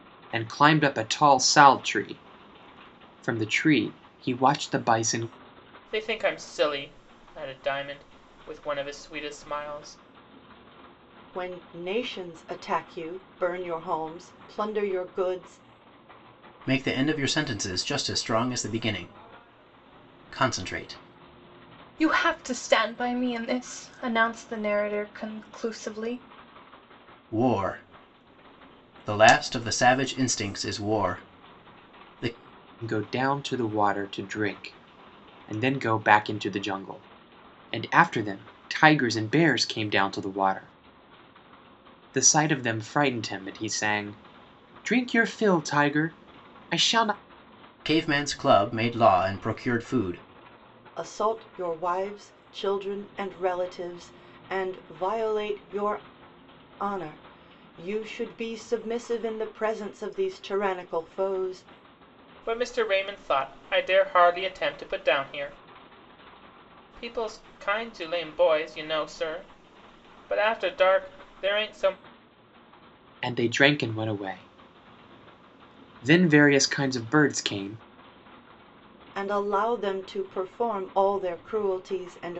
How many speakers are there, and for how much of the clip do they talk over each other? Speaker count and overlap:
five, no overlap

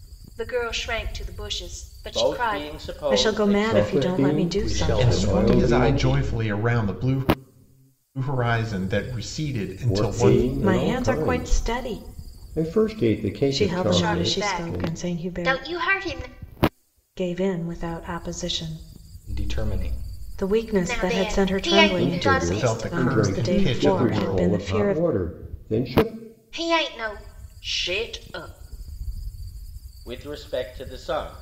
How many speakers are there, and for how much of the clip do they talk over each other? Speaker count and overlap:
six, about 39%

